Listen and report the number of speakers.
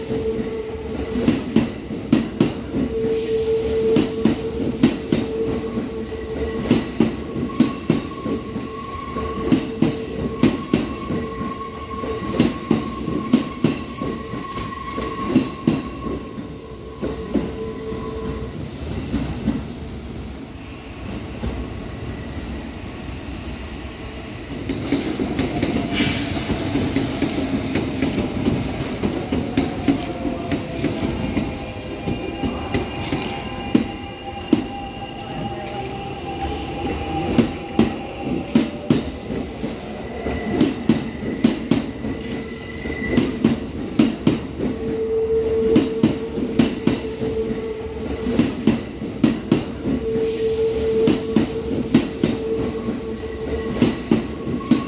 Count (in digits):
0